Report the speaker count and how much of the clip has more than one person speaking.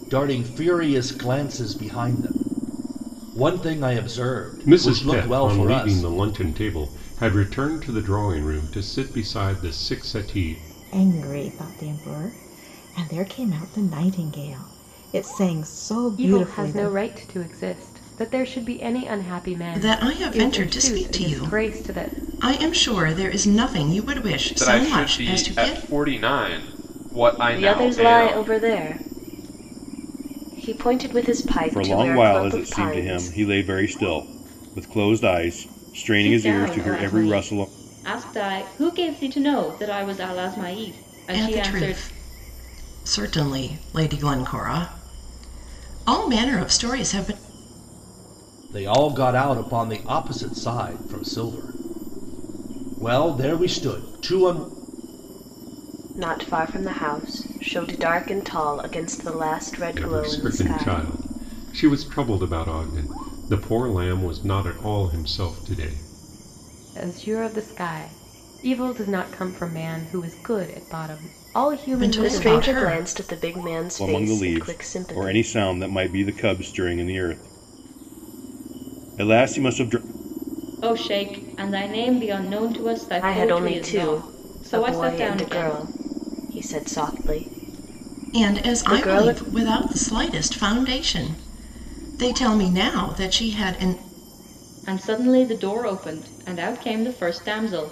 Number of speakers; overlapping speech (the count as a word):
nine, about 18%